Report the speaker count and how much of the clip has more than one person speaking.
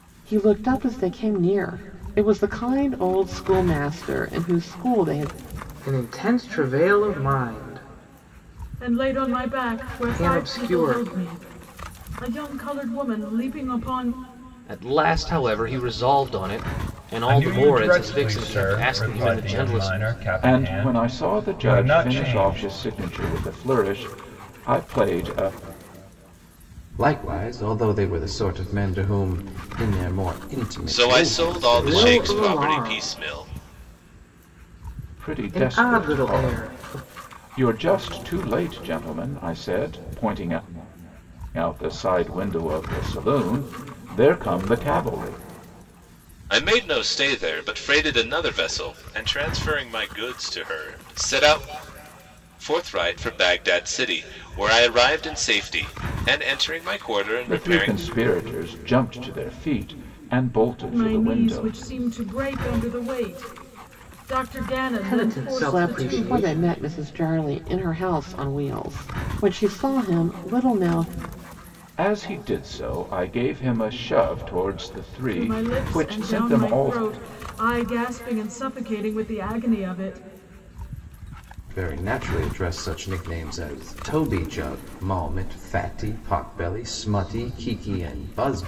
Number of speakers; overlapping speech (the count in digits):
8, about 19%